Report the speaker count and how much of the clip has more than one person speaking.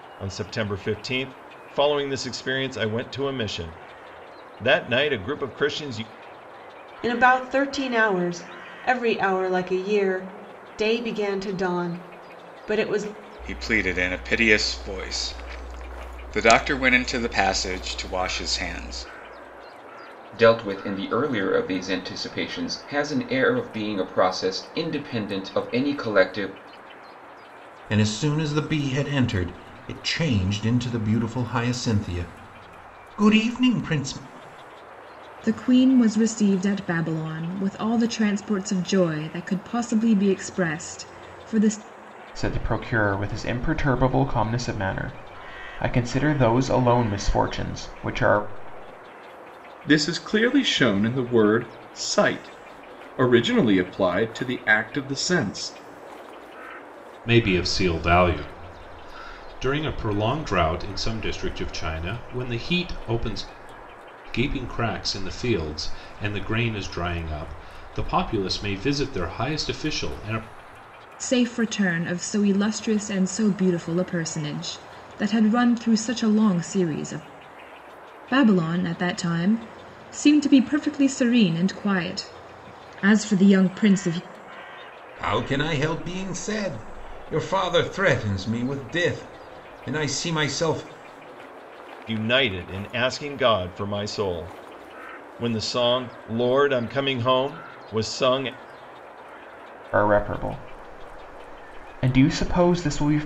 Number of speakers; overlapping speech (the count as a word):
nine, no overlap